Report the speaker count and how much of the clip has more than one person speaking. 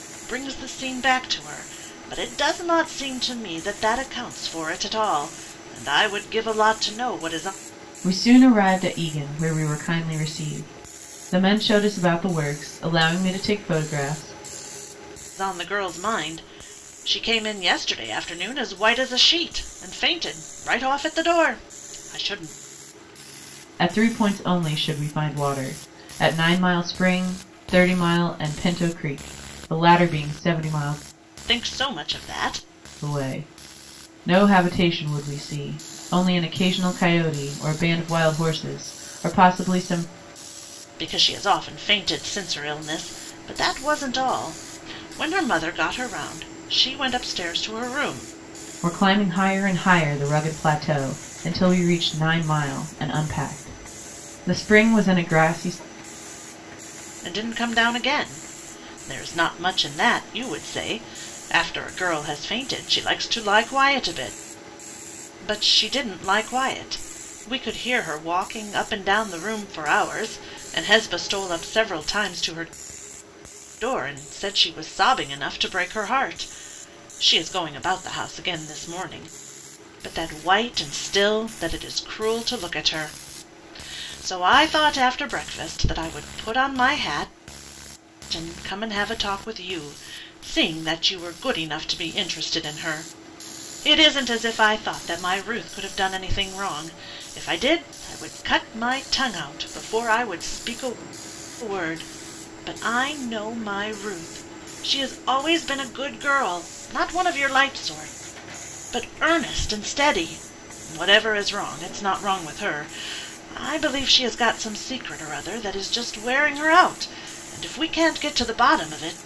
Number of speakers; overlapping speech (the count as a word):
two, no overlap